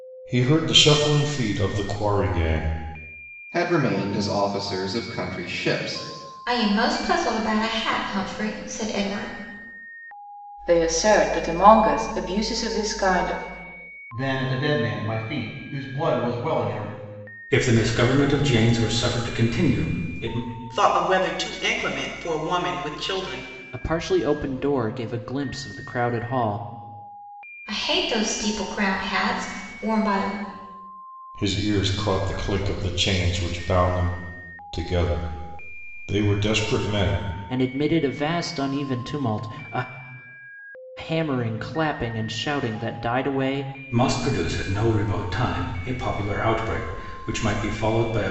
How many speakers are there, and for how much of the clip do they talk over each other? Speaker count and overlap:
8, no overlap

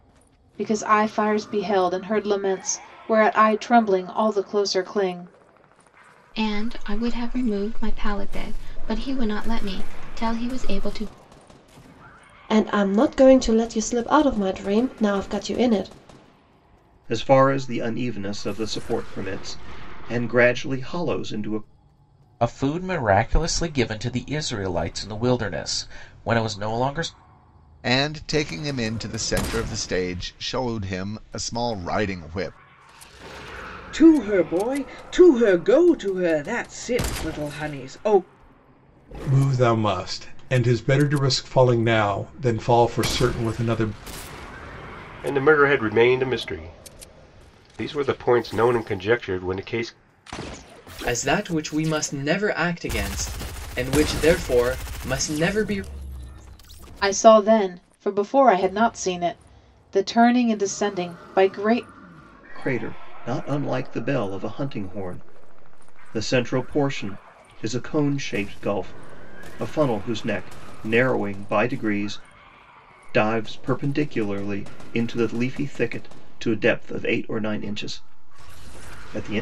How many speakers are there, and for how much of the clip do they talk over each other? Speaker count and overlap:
10, no overlap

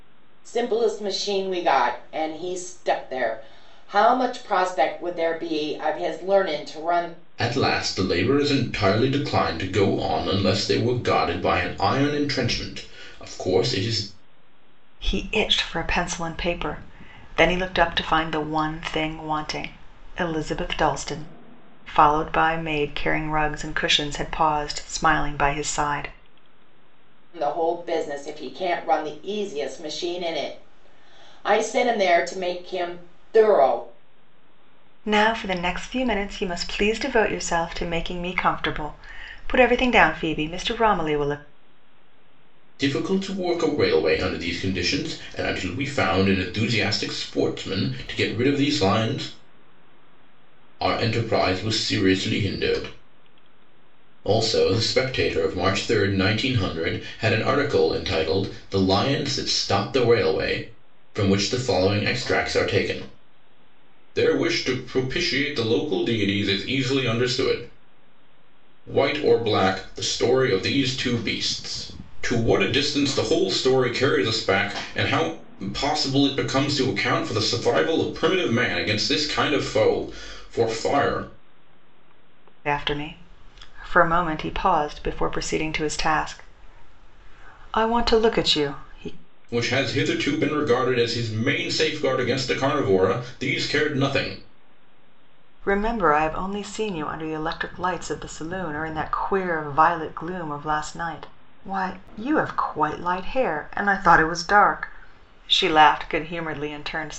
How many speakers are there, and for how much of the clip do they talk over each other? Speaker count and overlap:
3, no overlap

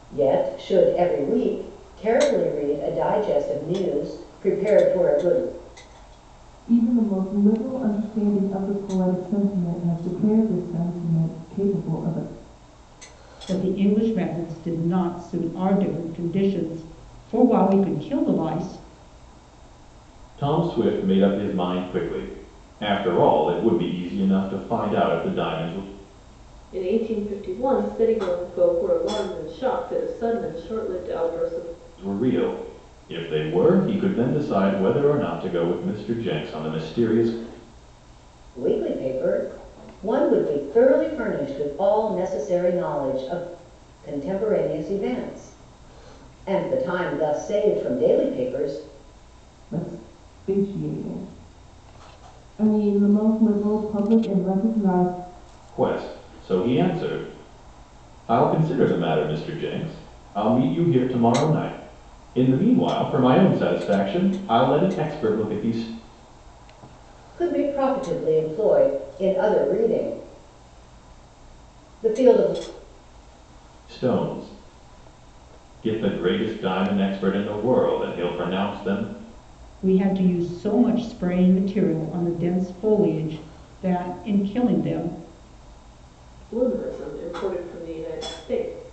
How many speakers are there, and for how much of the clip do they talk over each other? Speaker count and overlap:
5, no overlap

